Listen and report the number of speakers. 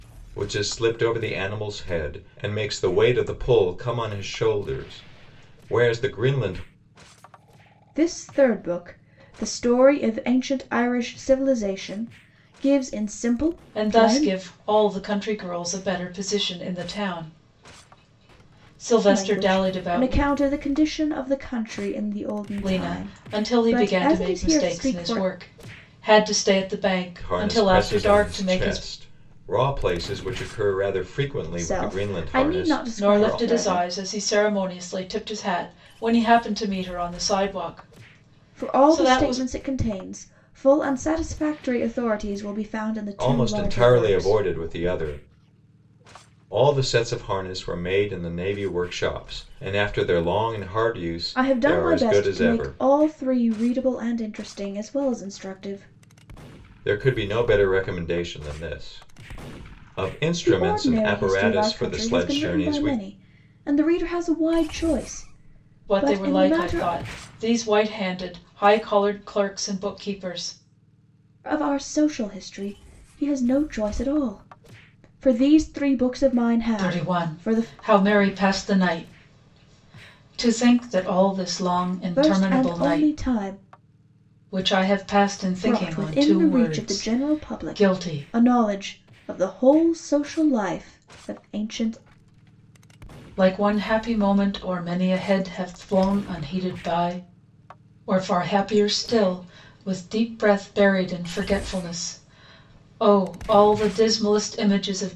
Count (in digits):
3